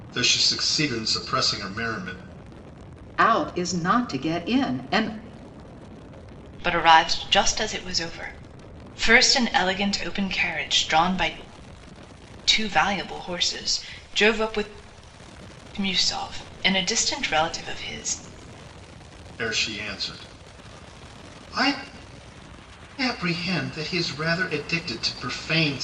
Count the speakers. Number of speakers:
3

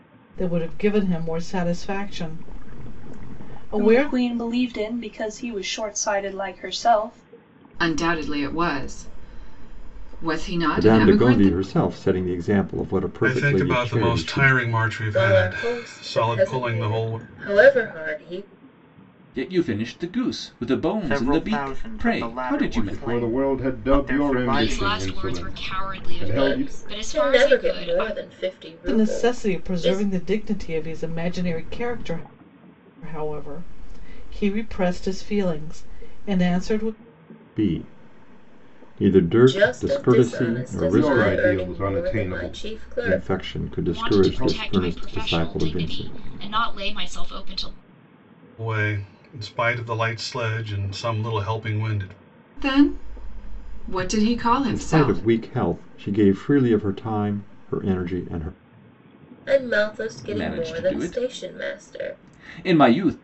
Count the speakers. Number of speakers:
10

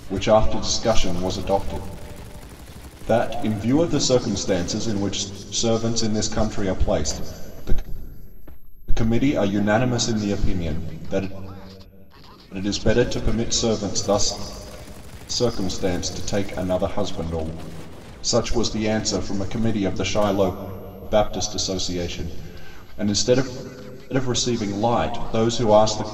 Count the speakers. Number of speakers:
1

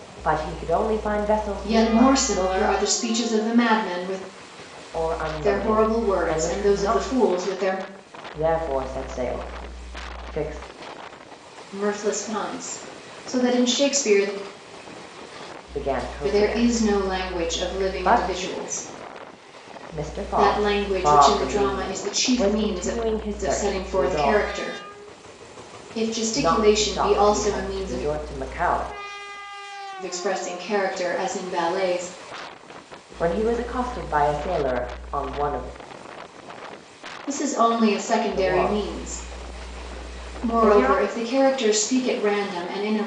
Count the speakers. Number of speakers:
2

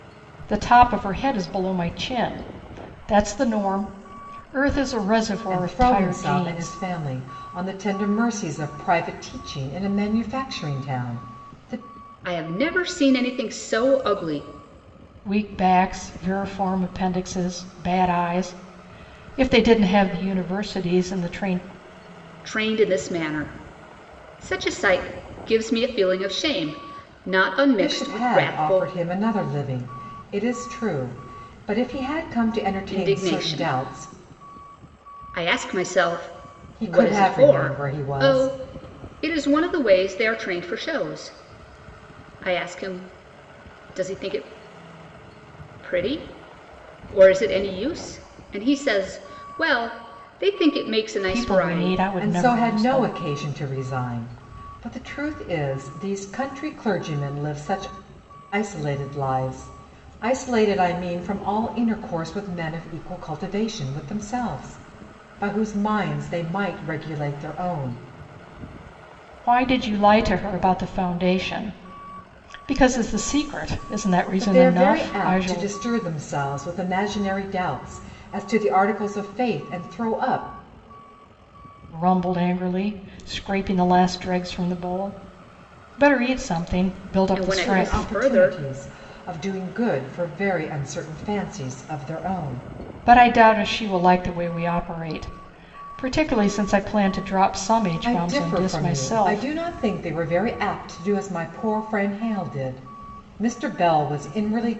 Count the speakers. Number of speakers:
3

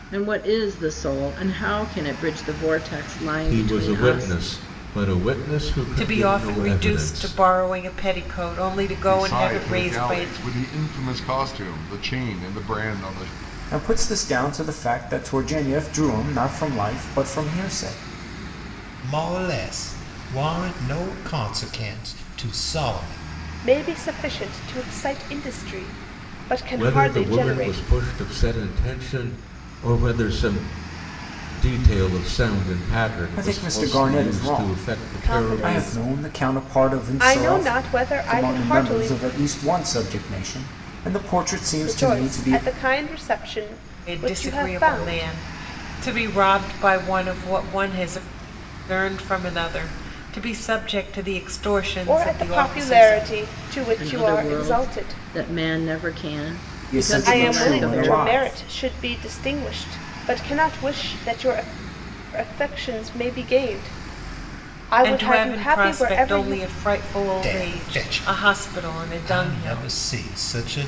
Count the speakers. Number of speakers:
7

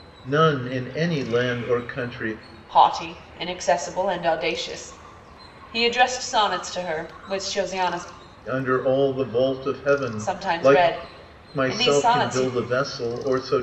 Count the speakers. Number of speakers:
2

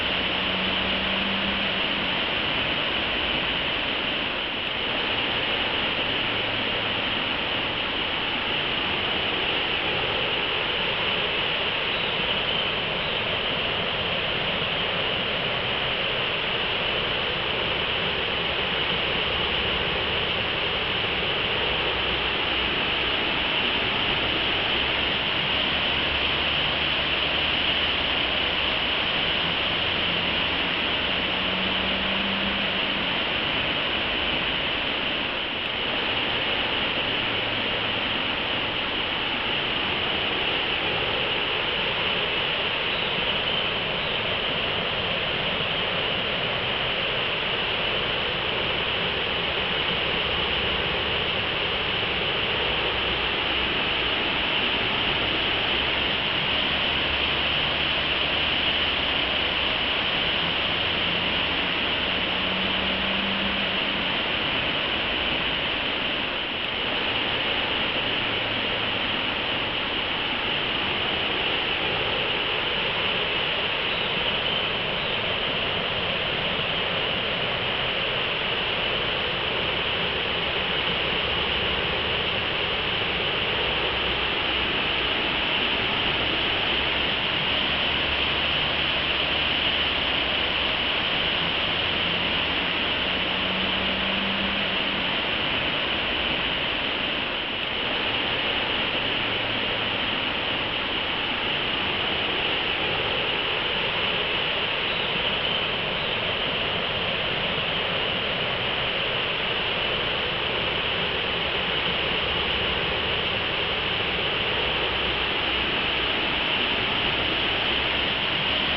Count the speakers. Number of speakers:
0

